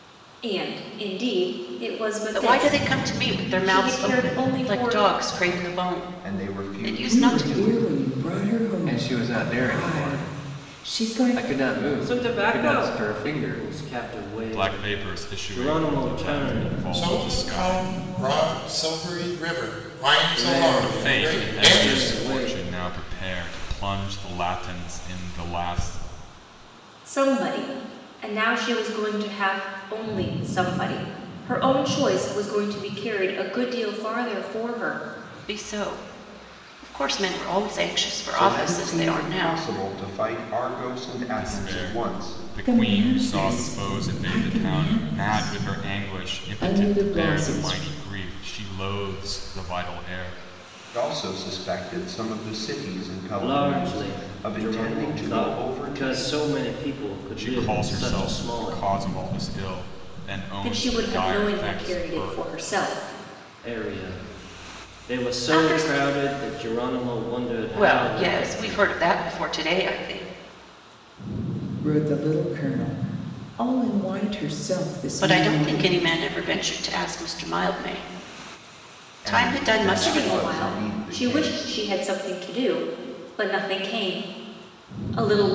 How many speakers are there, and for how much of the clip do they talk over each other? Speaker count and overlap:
8, about 41%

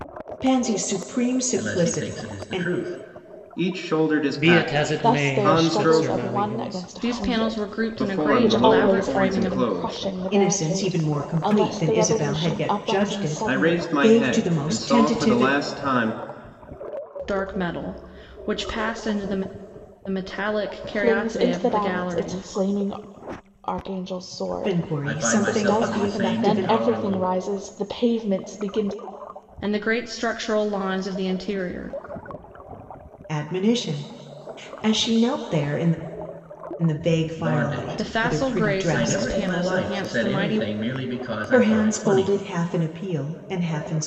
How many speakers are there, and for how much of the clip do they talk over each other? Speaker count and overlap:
6, about 45%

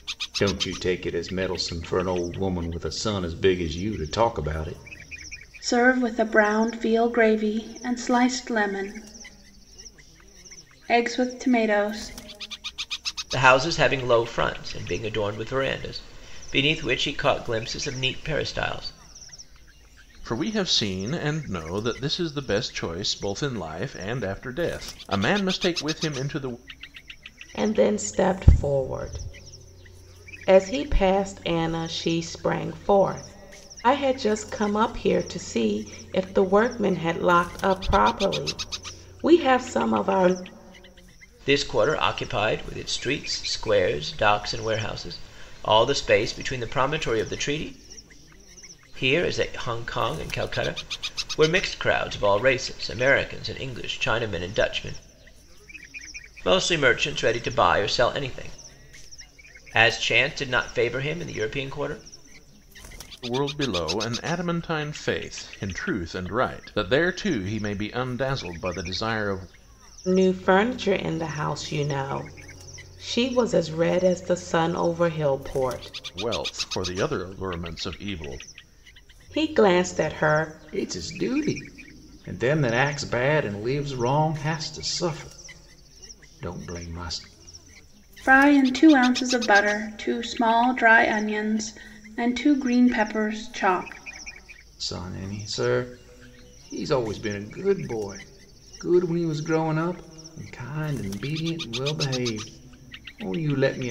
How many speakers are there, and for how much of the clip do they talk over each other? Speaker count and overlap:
5, no overlap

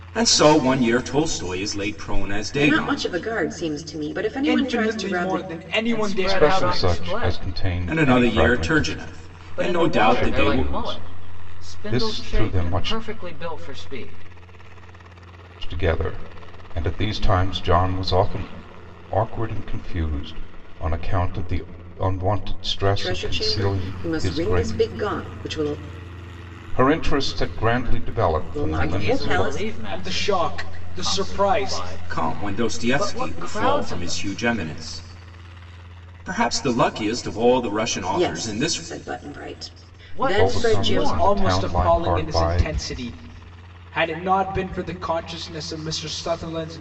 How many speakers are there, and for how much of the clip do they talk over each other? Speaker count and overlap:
5, about 40%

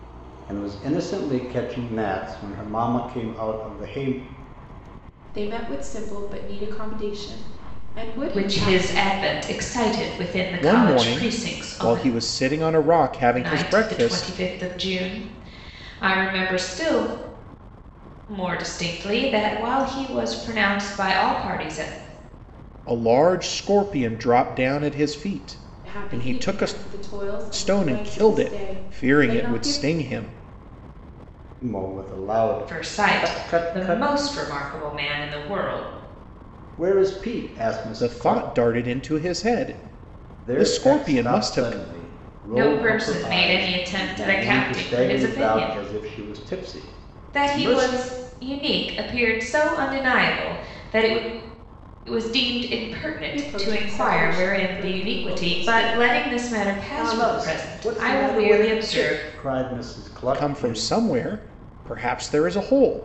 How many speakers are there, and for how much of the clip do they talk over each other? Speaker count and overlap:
4, about 31%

